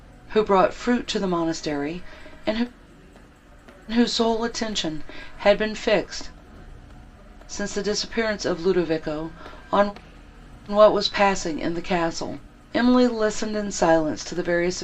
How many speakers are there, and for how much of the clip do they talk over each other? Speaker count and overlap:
one, no overlap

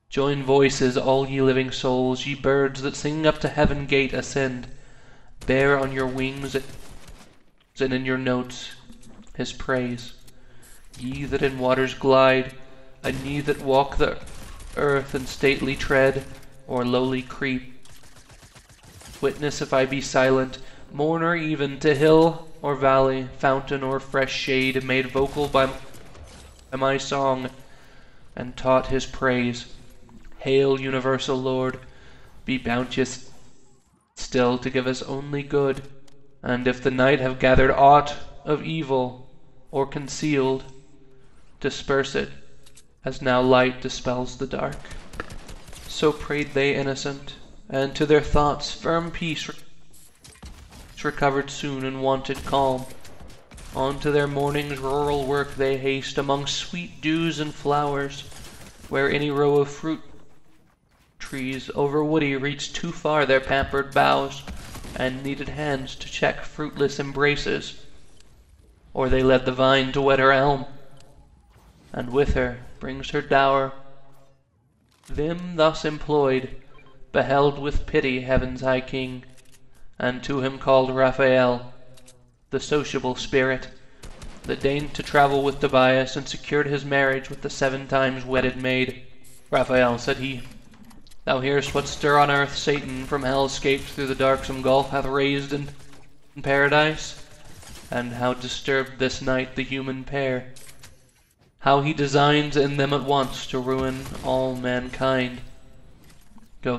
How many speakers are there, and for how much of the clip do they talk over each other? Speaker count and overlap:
one, no overlap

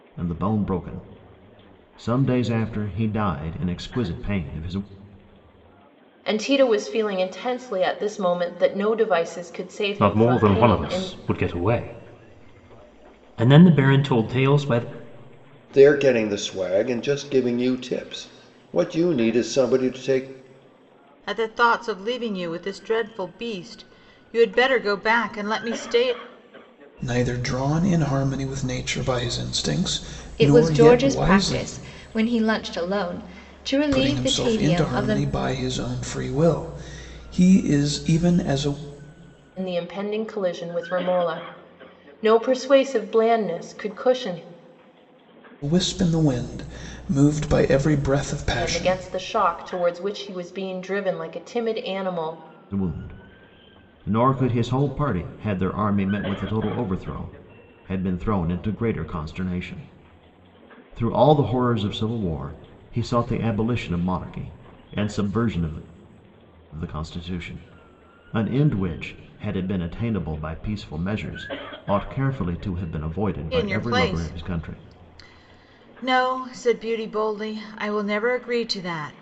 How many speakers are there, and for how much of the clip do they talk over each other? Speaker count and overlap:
seven, about 7%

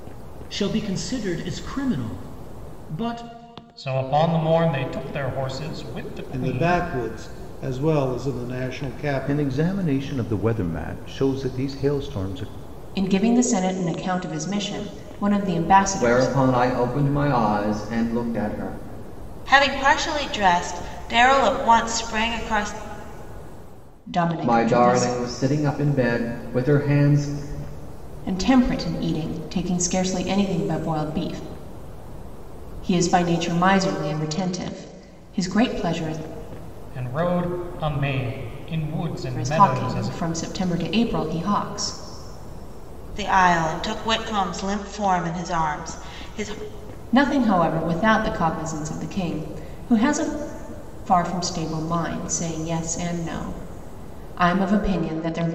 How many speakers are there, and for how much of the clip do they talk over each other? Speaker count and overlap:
seven, about 5%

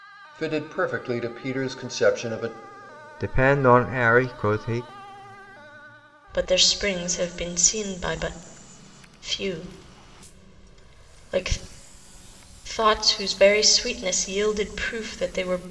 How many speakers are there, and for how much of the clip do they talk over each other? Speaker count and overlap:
three, no overlap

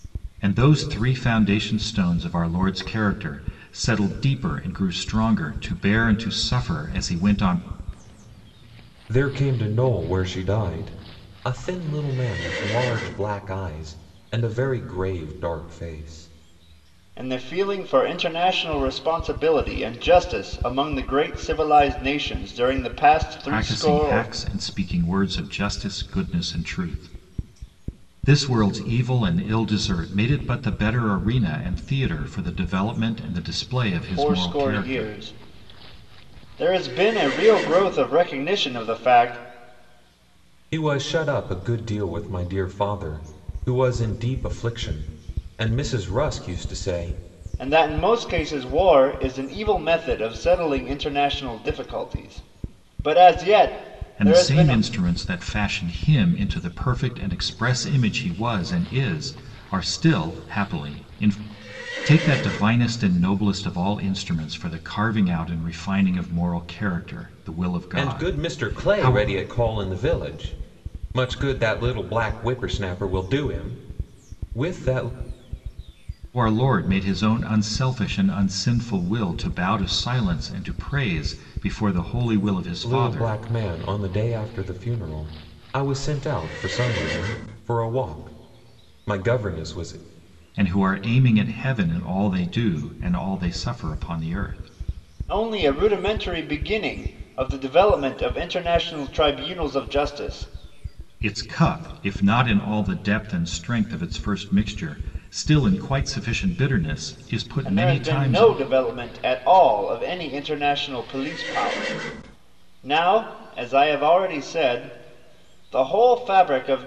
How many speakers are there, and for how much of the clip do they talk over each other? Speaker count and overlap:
three, about 5%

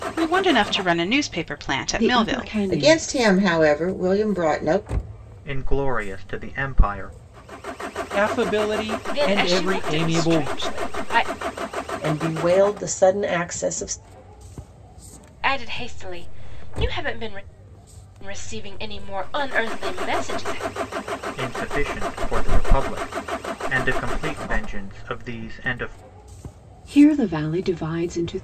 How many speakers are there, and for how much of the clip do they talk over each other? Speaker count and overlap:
seven, about 9%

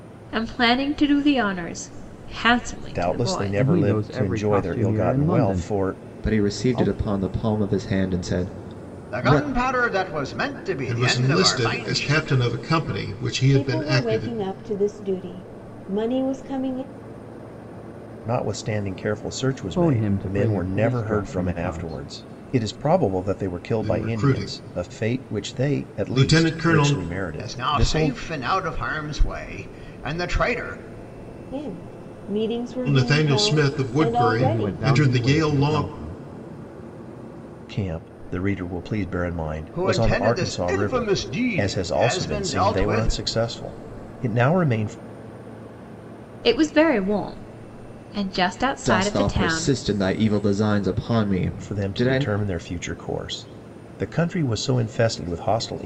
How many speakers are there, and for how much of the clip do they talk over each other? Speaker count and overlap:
seven, about 38%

